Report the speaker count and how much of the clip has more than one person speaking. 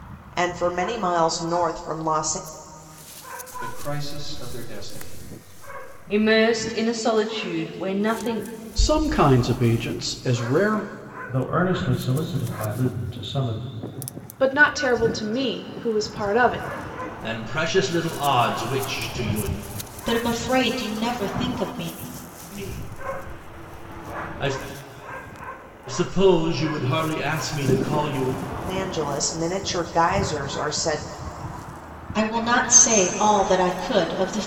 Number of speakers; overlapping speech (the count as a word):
eight, no overlap